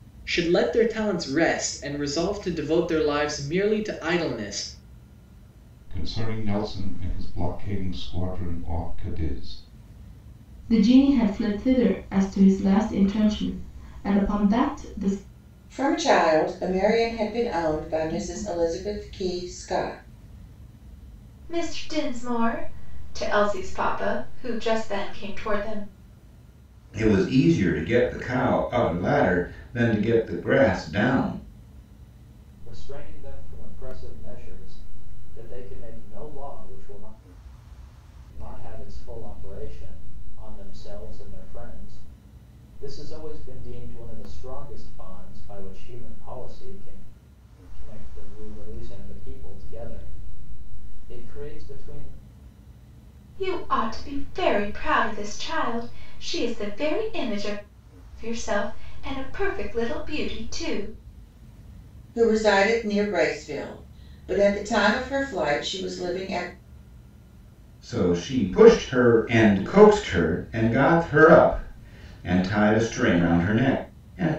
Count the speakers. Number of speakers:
seven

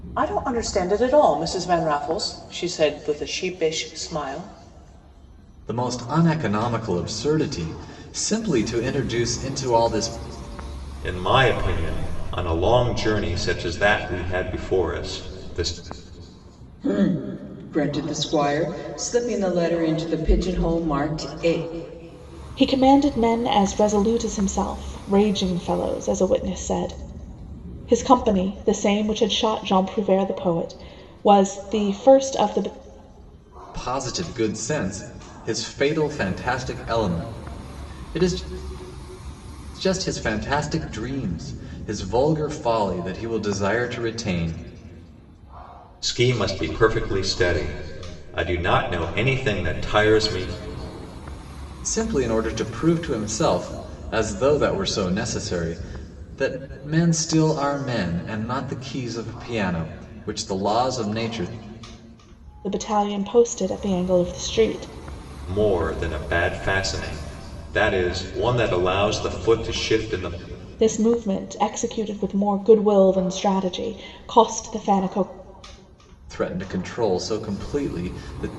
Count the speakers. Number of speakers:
five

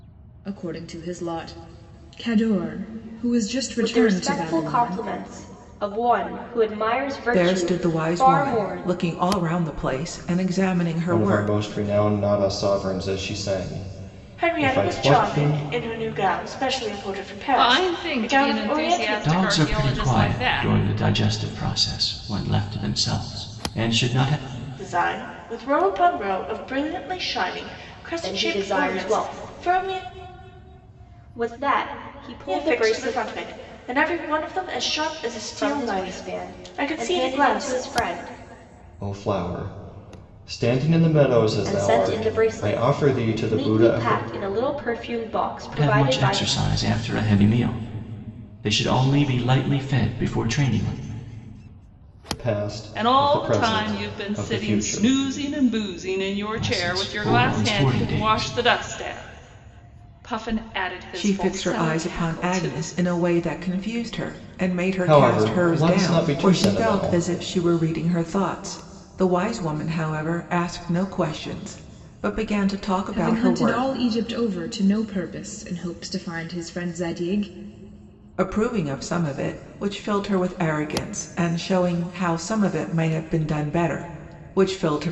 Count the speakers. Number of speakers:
seven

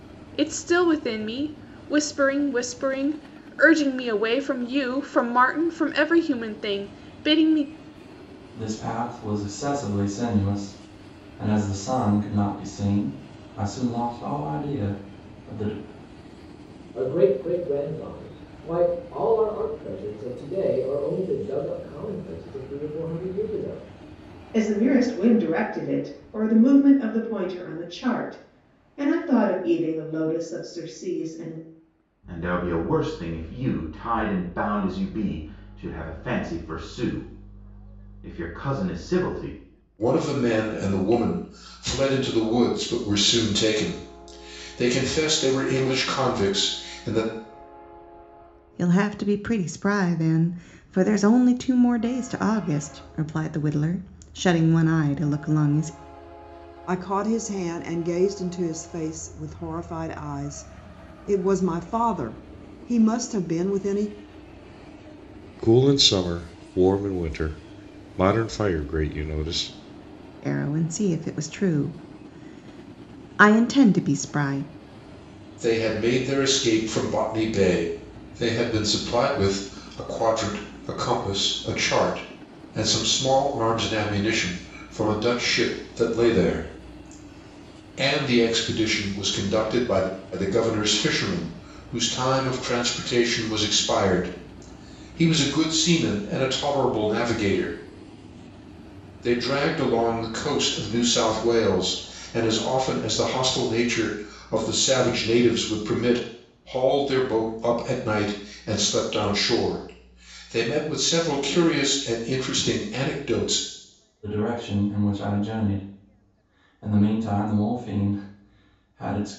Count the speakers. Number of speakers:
nine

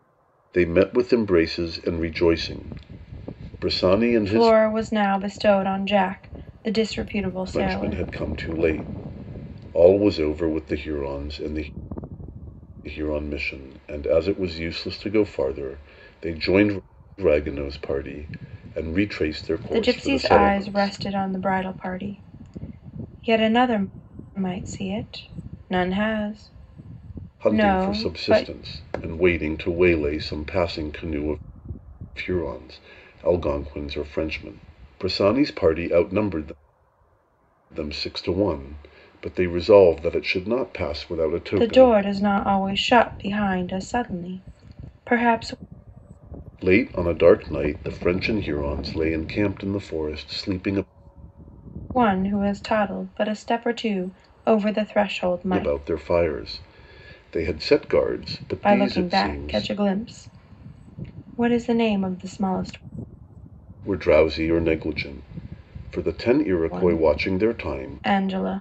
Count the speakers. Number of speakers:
two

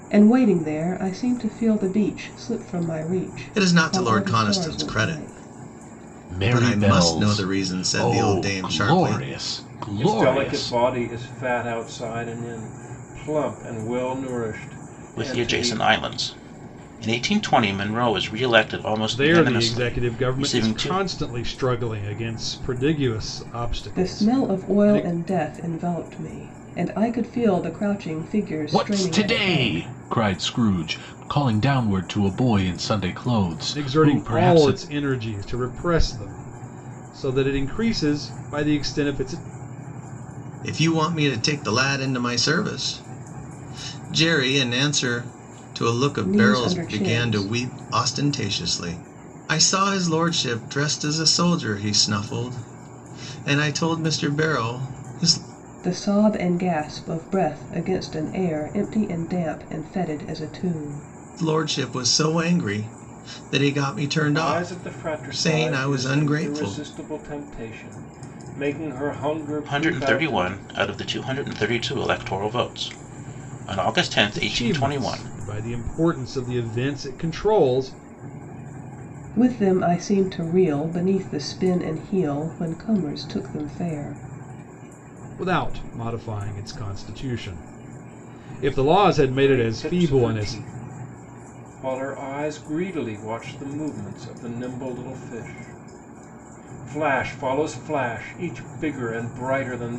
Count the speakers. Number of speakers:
six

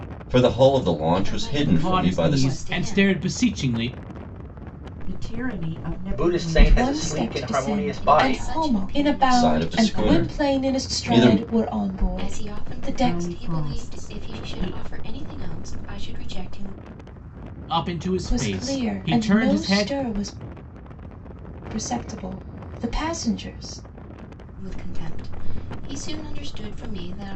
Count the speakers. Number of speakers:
six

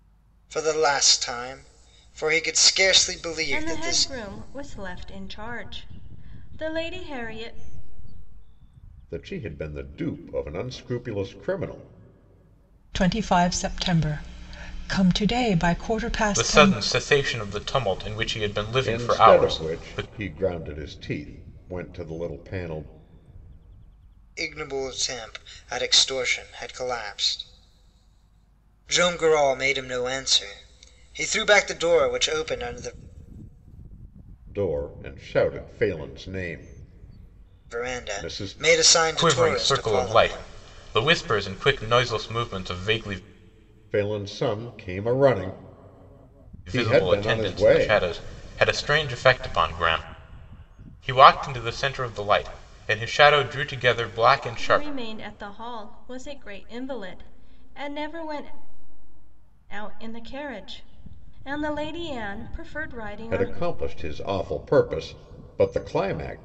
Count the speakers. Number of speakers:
five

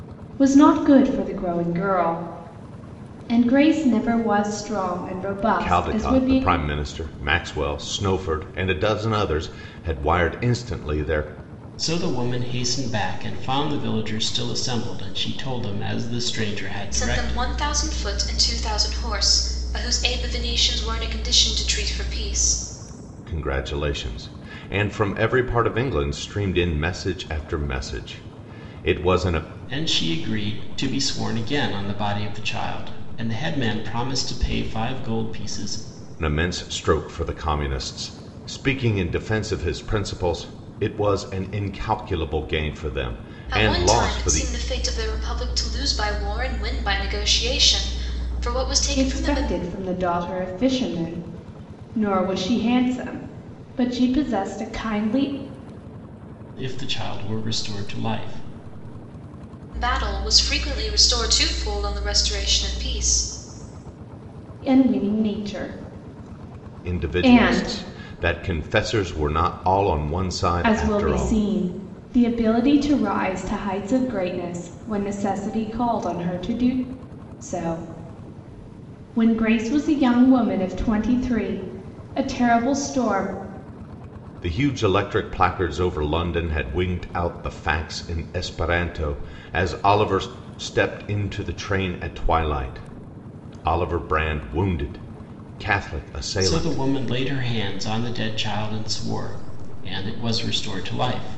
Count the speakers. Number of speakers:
four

